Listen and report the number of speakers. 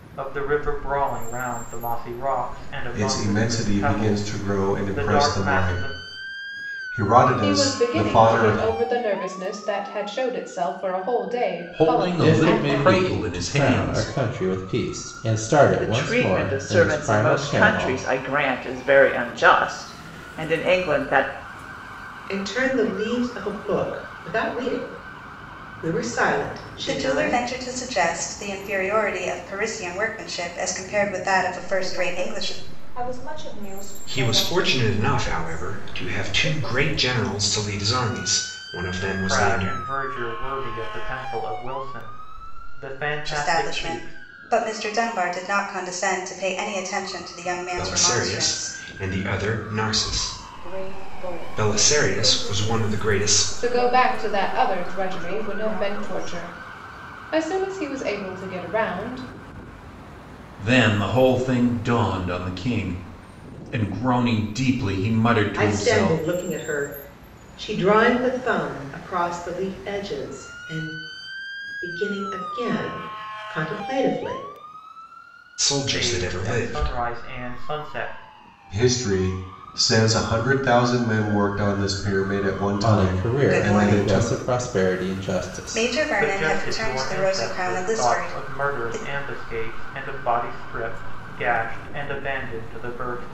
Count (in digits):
10